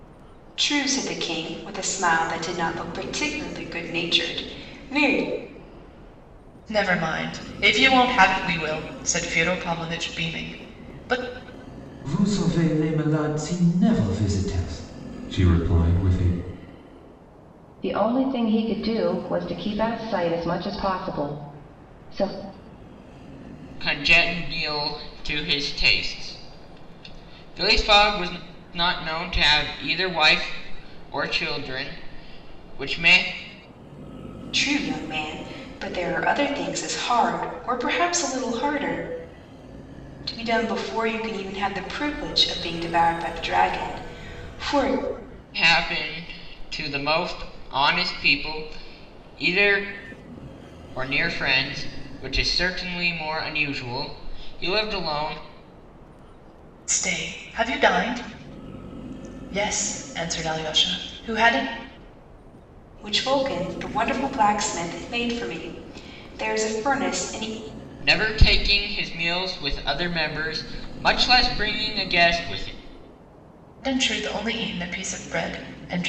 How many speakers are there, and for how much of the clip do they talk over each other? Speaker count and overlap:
5, no overlap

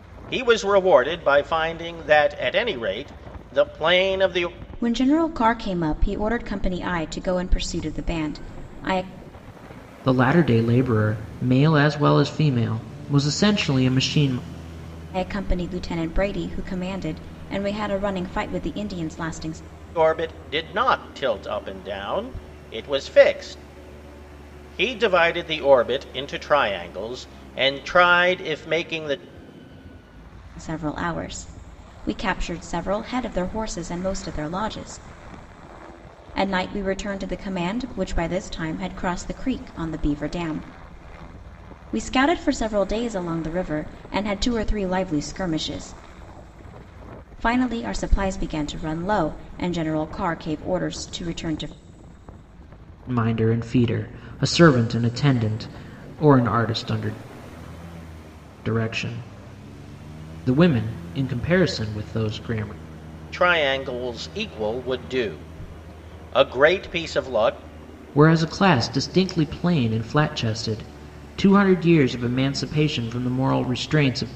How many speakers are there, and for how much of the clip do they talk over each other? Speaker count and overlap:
3, no overlap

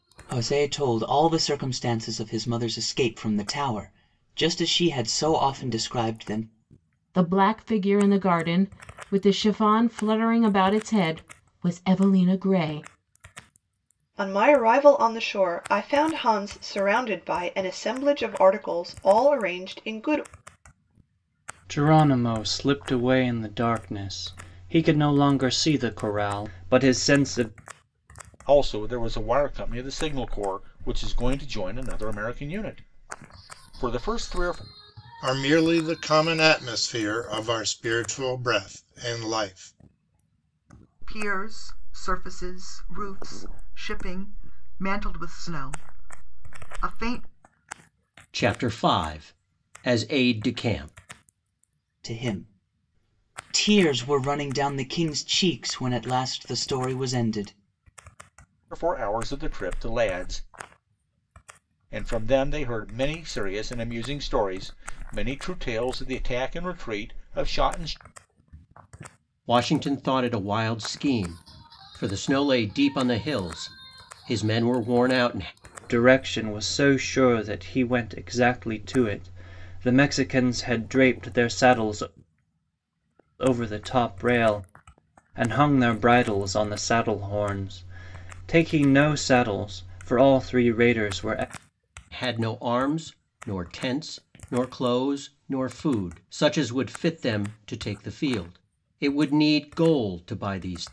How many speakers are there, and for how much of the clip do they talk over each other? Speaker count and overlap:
8, no overlap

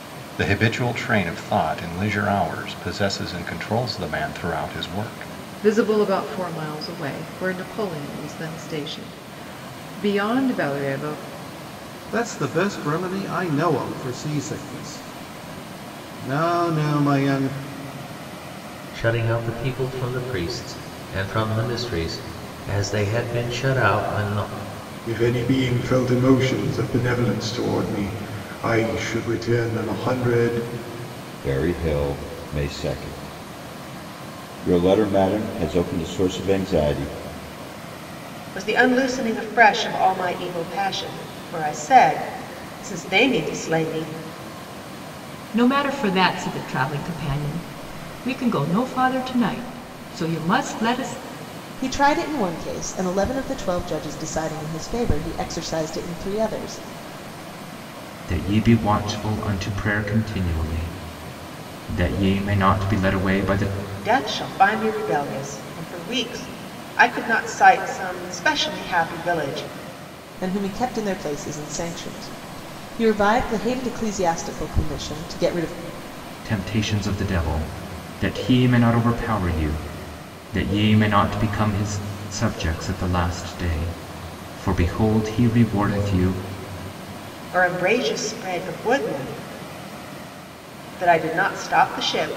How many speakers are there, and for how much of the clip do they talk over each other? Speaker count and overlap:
10, no overlap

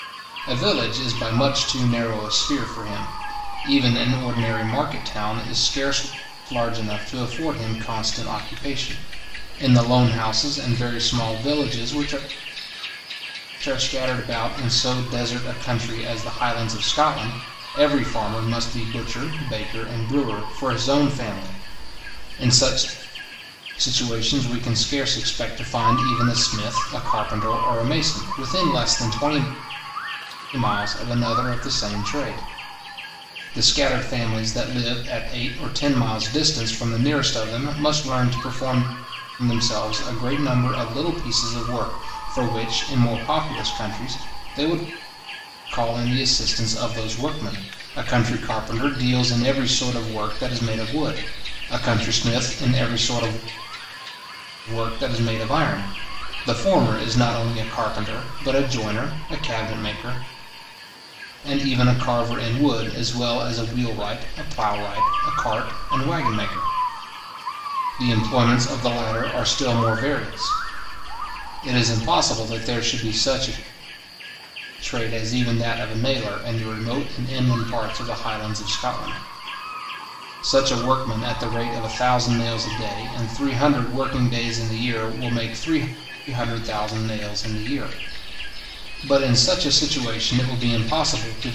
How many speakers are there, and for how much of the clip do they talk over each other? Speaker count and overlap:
1, no overlap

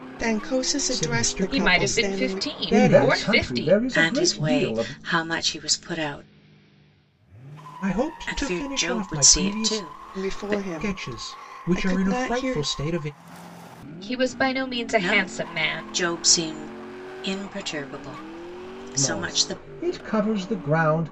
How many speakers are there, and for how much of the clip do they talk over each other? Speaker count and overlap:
5, about 46%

